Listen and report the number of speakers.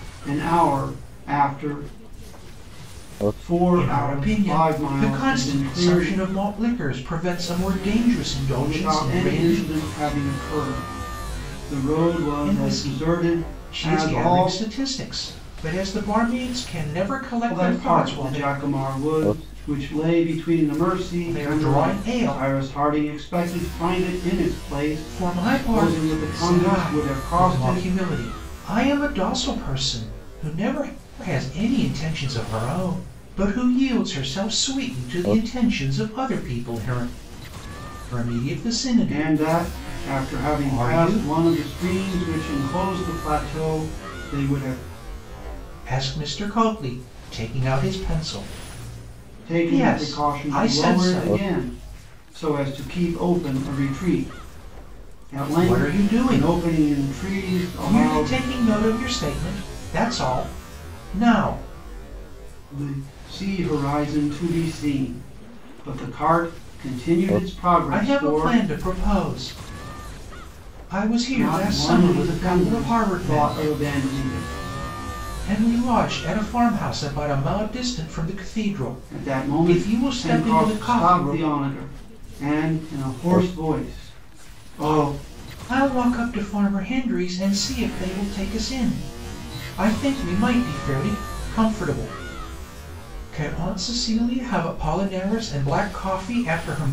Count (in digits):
2